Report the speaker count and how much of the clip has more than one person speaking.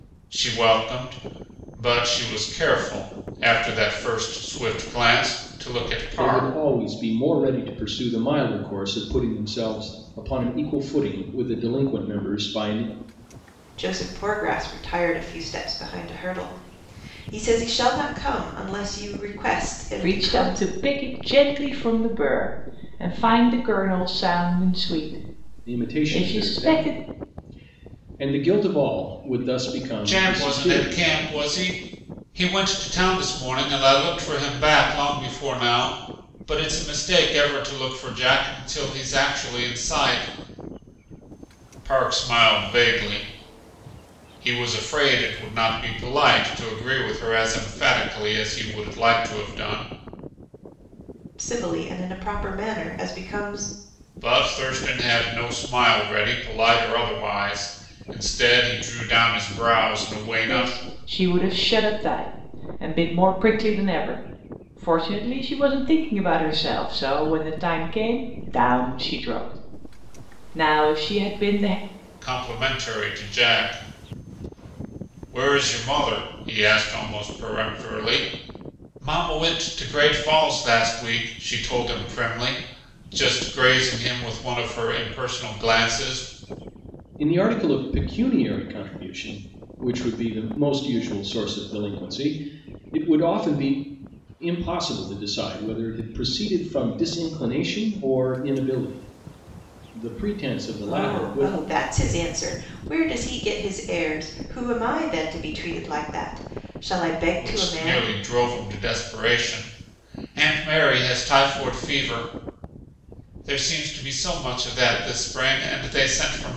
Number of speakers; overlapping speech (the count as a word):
four, about 5%